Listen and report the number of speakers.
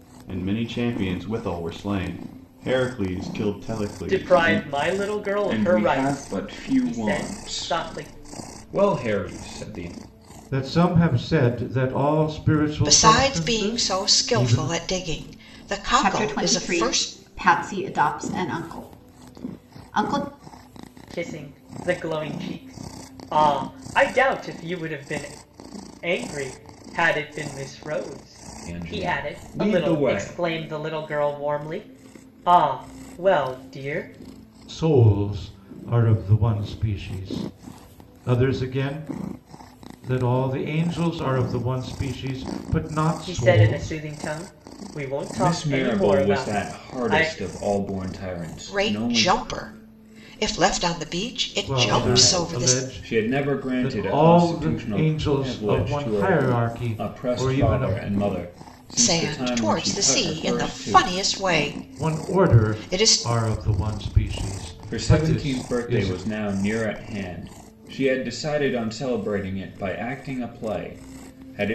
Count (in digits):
6